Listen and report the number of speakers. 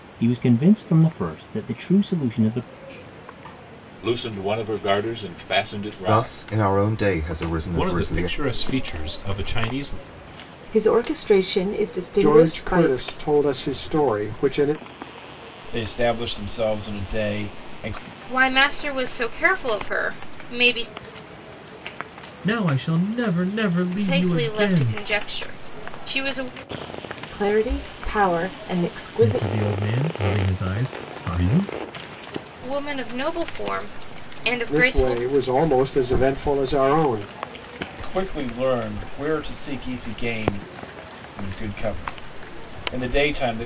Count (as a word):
nine